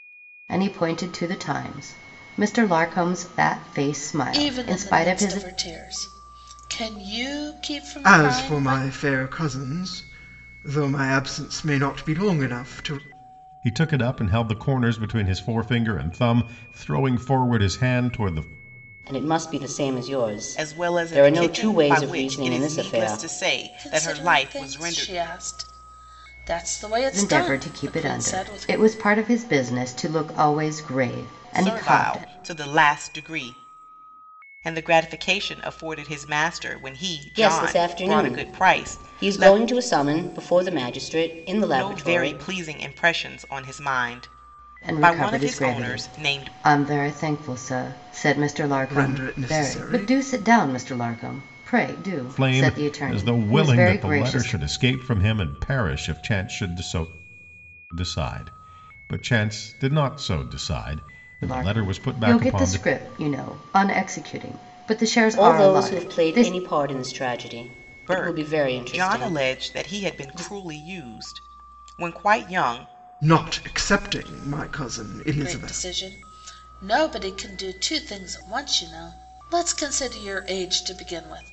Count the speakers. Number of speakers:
6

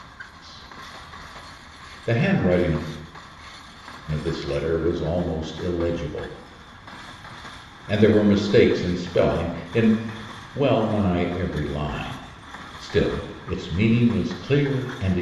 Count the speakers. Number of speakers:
1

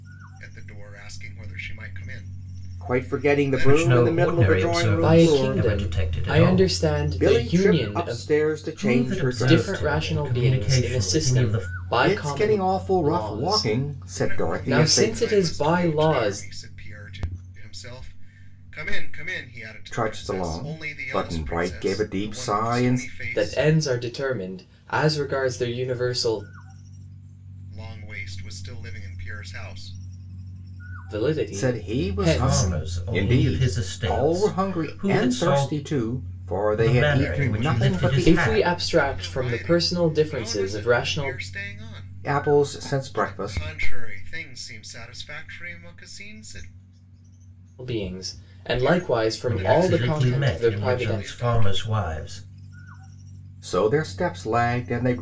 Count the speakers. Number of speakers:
4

